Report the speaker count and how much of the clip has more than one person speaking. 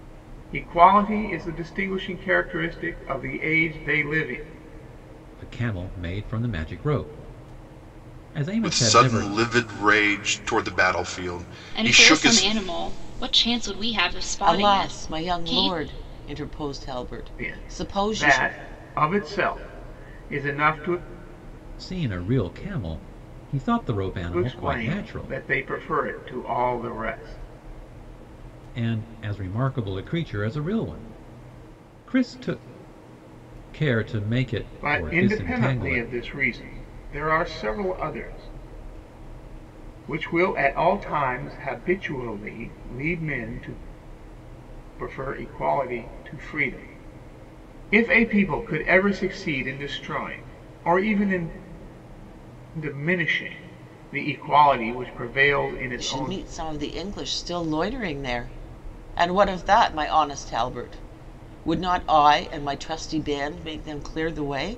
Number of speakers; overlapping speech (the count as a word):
five, about 10%